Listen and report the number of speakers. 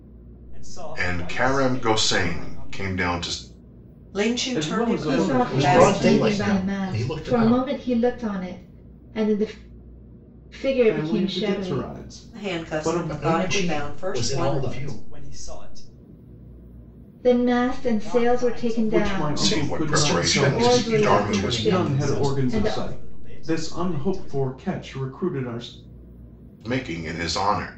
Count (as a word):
six